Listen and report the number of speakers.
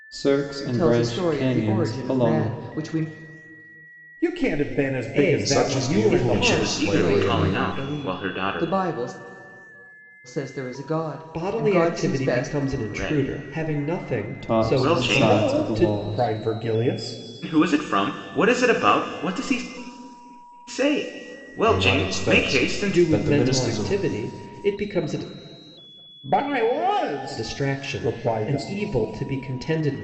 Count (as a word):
six